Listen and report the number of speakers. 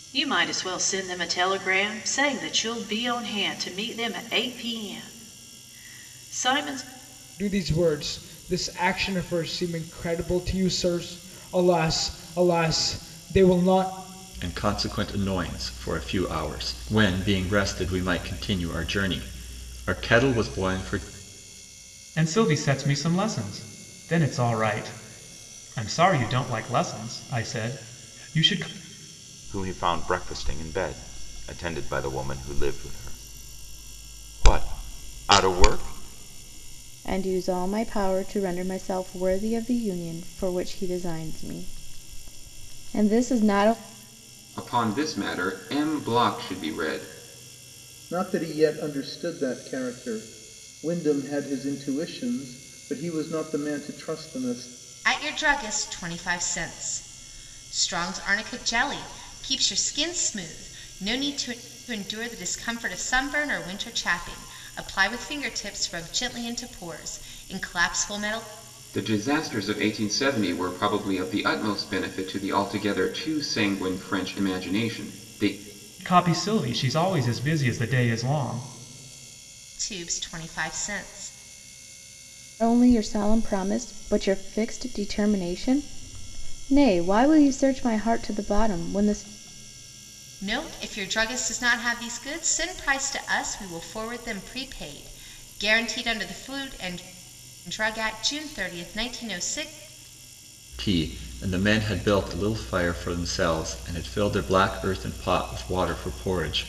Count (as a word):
nine